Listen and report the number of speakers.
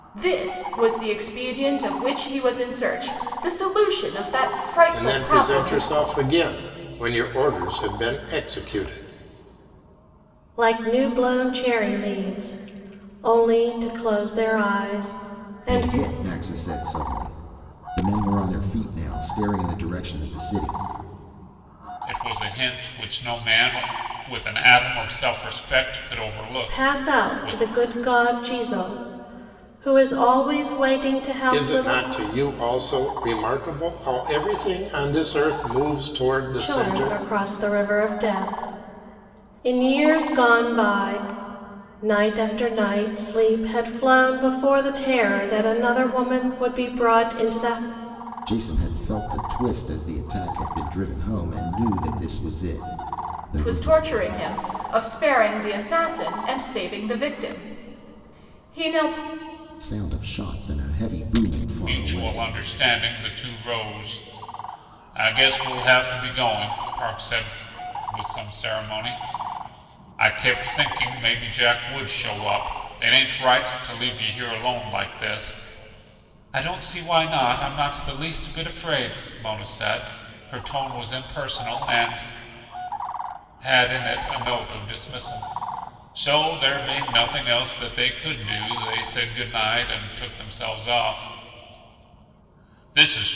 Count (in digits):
5